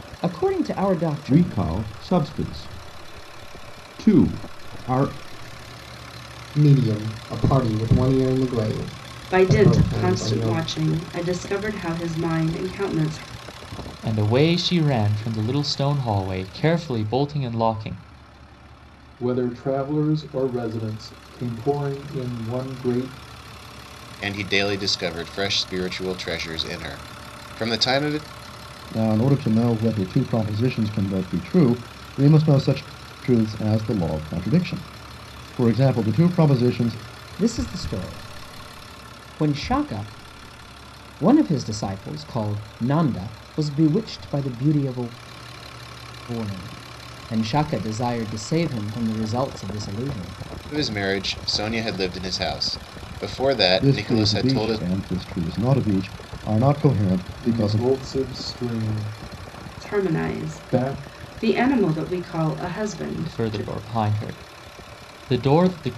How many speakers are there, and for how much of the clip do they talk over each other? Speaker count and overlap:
eight, about 8%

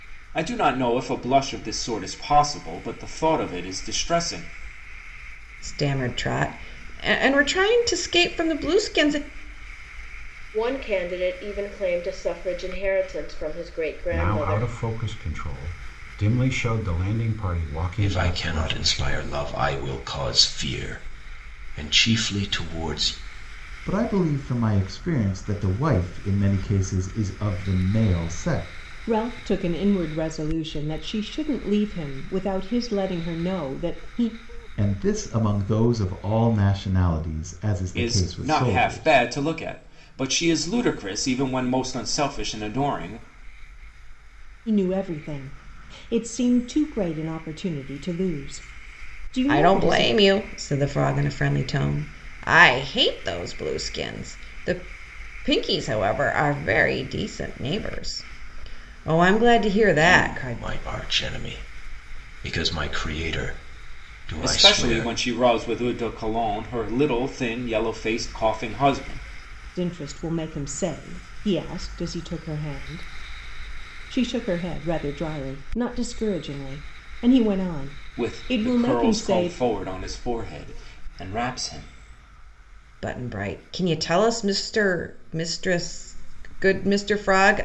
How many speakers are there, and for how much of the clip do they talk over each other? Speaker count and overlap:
seven, about 8%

